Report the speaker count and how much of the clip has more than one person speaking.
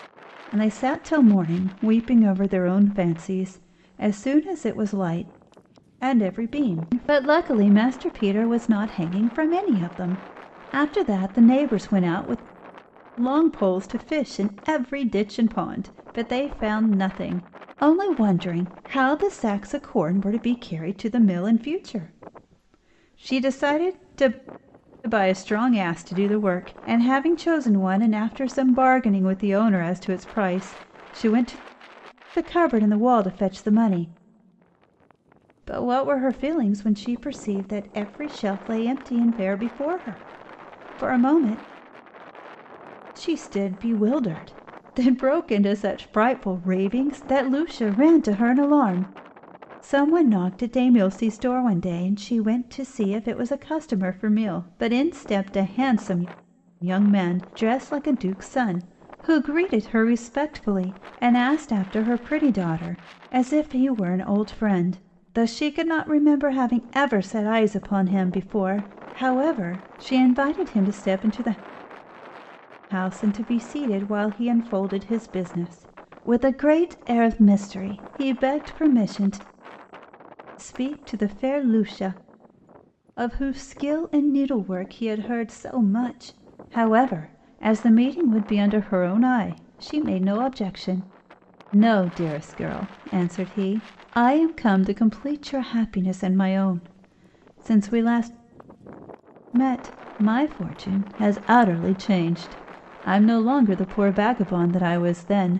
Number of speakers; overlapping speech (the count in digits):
1, no overlap